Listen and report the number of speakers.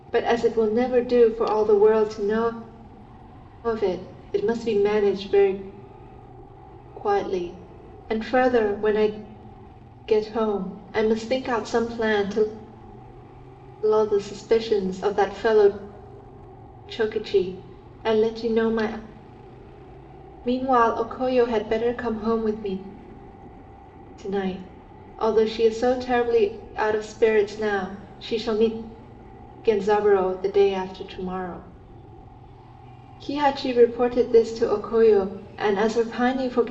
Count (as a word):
one